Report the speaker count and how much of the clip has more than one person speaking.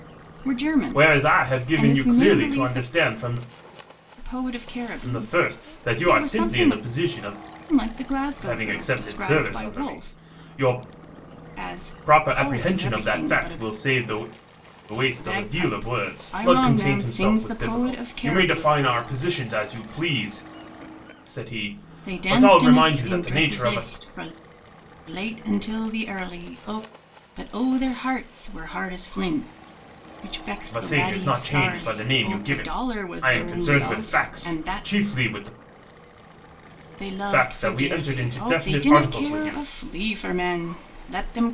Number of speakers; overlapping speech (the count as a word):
two, about 45%